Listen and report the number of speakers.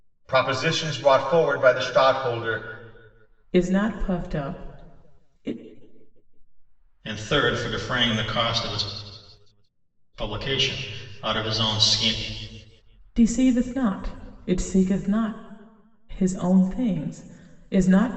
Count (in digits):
3